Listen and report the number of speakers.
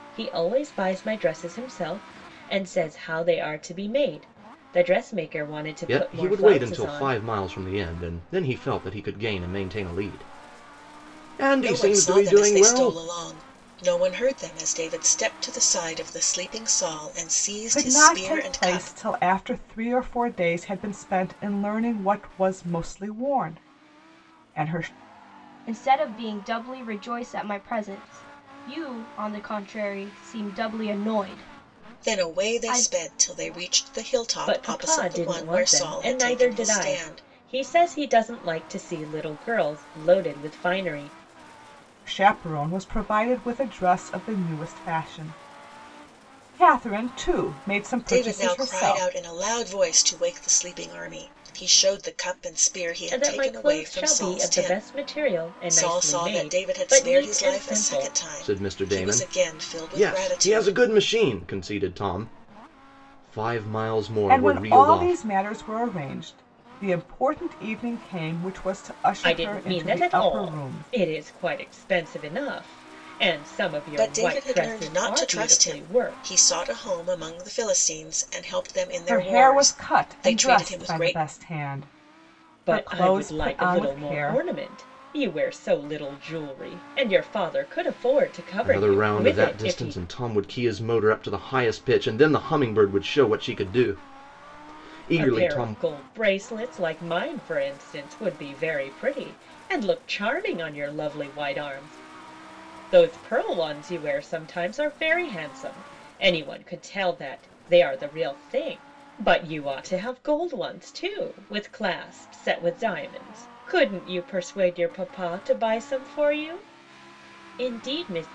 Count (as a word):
five